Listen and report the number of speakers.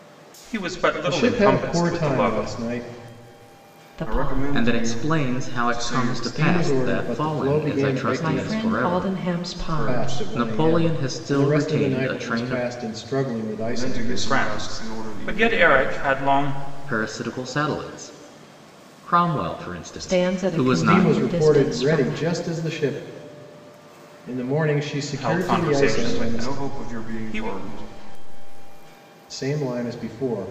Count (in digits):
5